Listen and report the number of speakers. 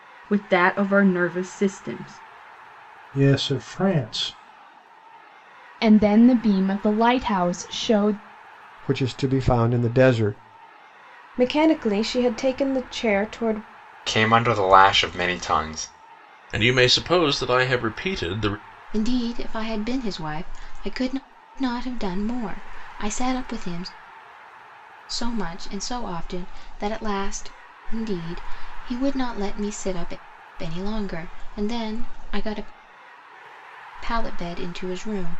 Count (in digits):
8